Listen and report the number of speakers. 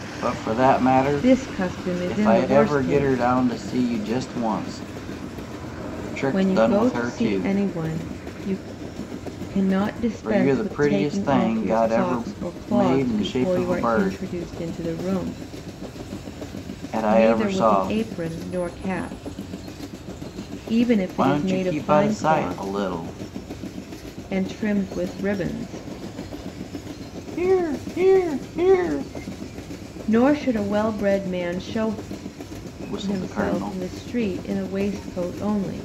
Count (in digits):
2